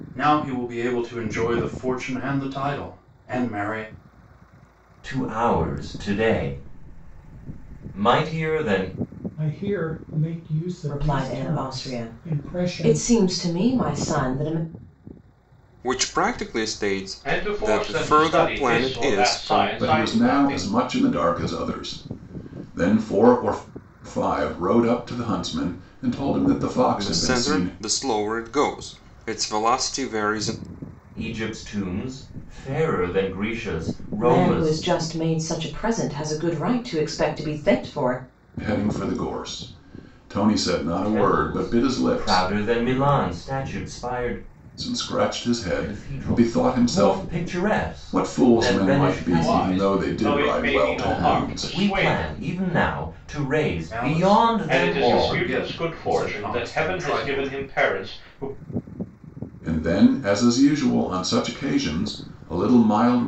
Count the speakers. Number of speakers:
seven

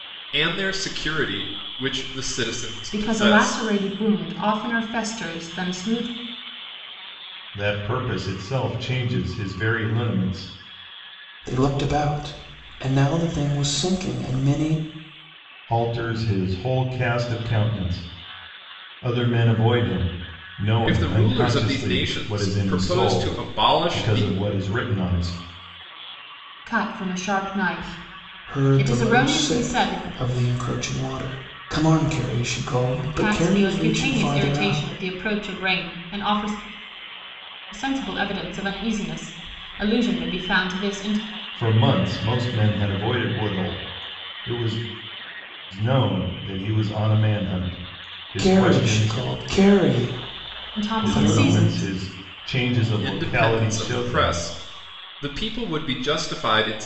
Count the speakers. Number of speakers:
four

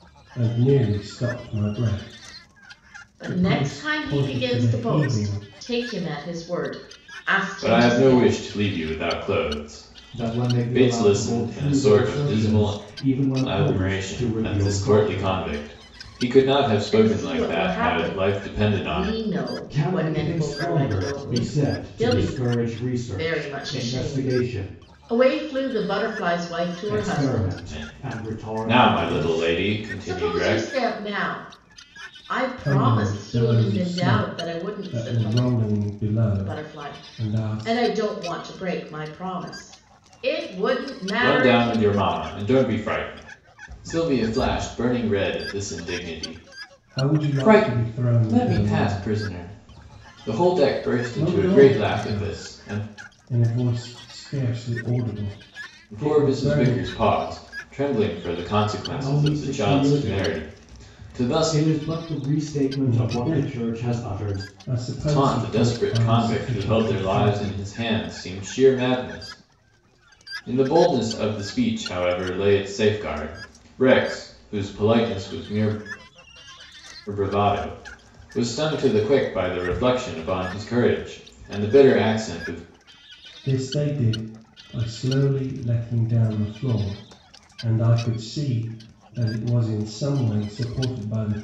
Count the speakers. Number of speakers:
four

